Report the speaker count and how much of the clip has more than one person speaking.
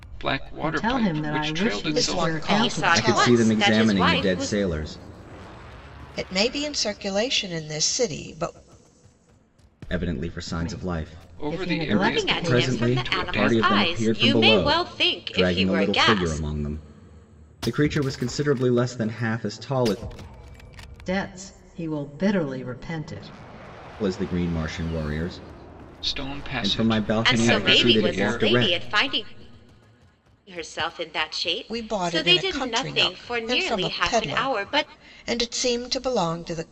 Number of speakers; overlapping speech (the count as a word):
five, about 41%